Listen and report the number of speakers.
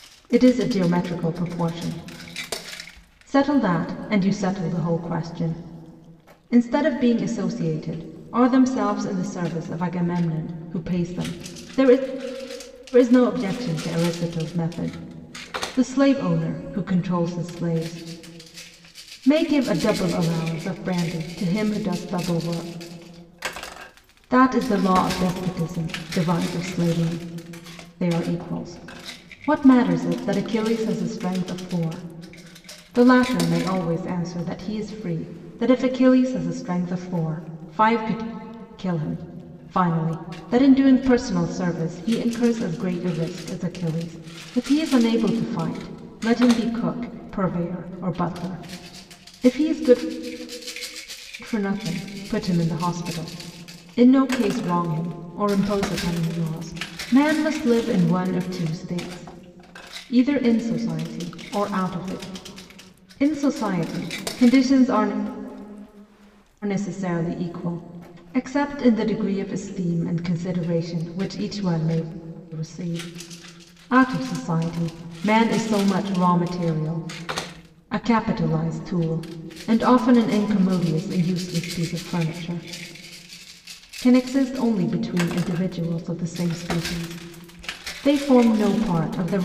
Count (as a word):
one